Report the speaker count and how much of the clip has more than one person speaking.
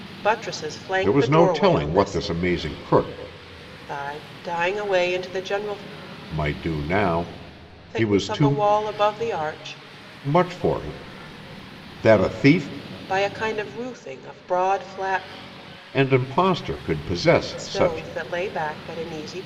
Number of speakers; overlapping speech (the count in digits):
2, about 13%